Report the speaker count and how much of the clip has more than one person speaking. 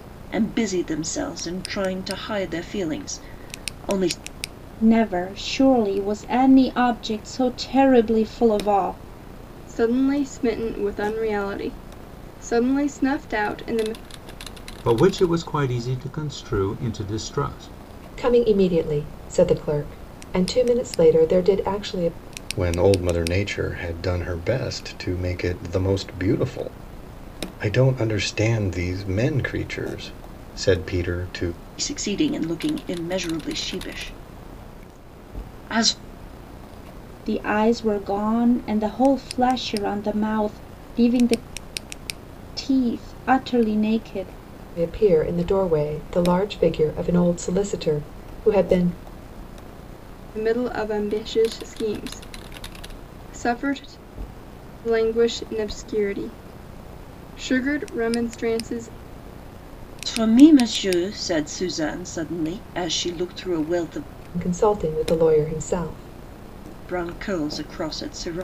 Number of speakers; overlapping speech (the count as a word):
six, no overlap